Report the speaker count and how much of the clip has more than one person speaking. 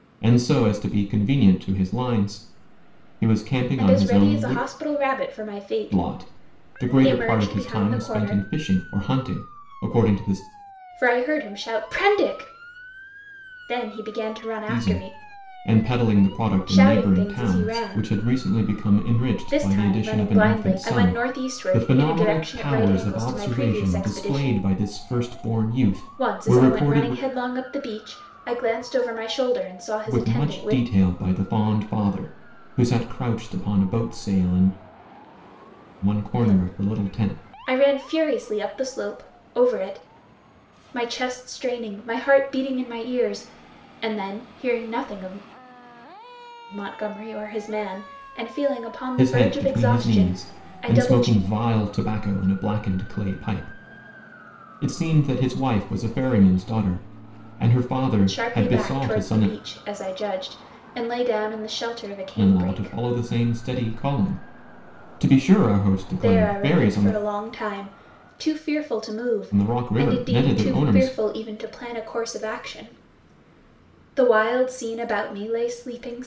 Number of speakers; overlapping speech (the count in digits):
2, about 28%